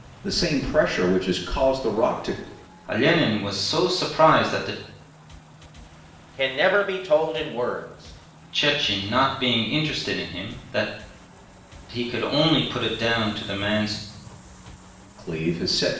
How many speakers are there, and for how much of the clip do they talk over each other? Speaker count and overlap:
3, no overlap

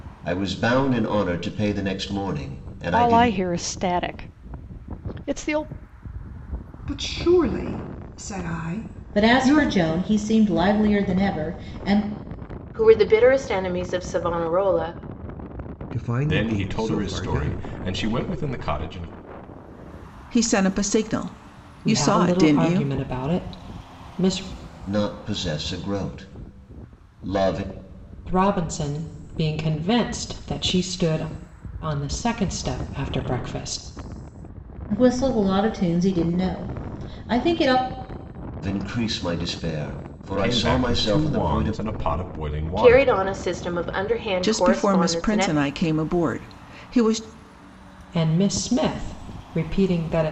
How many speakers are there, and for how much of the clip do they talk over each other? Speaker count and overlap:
9, about 13%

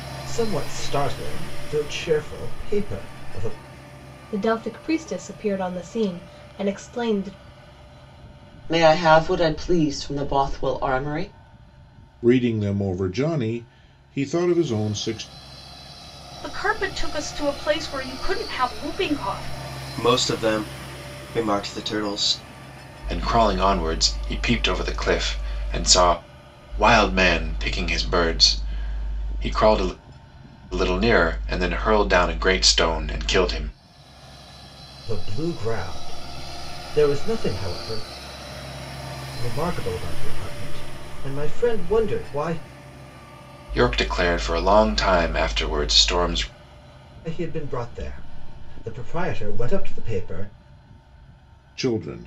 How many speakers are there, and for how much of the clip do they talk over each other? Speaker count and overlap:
7, no overlap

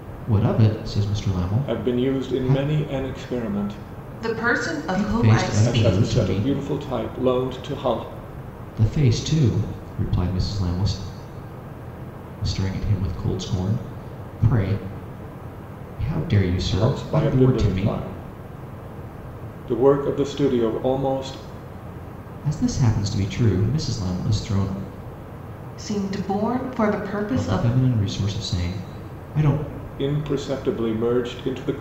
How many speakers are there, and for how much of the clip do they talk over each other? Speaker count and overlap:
3, about 13%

